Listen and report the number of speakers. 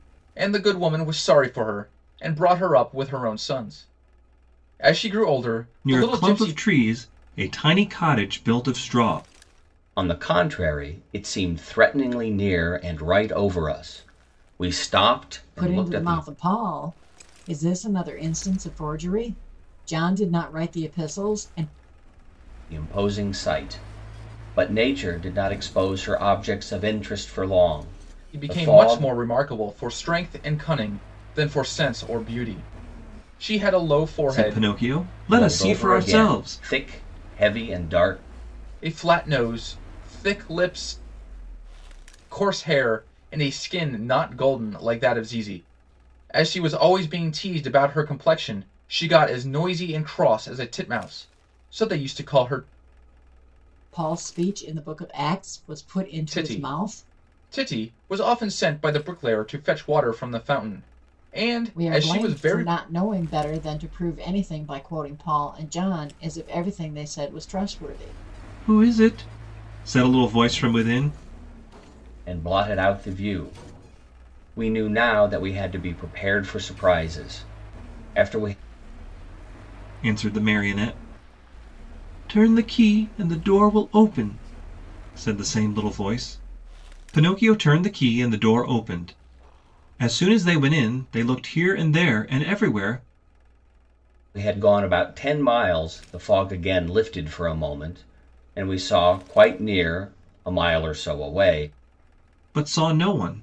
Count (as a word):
four